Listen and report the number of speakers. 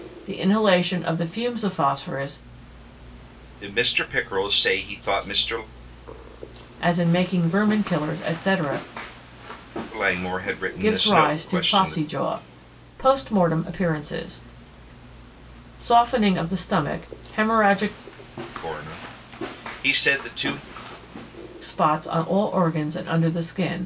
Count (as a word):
two